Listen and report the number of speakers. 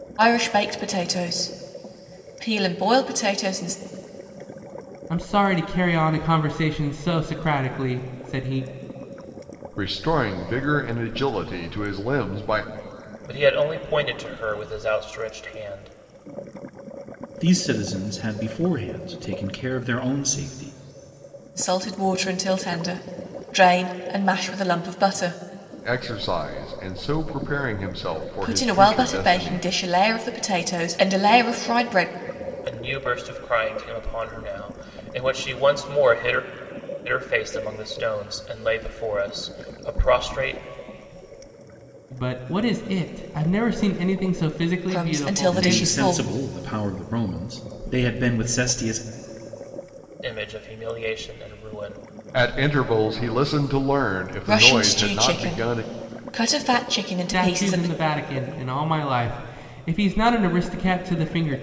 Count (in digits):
5